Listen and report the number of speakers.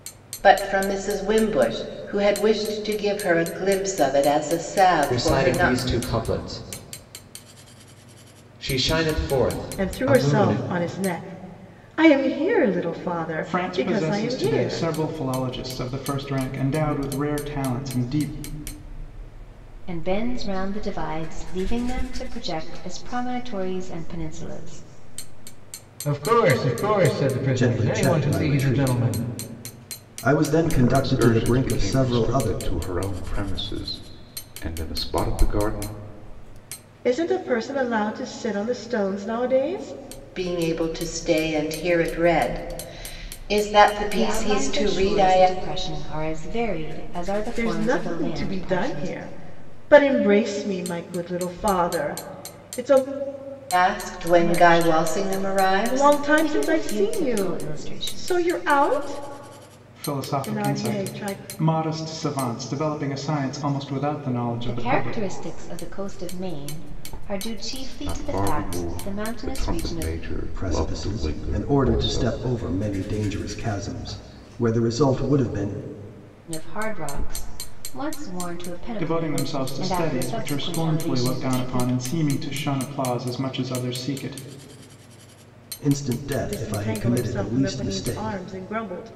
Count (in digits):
8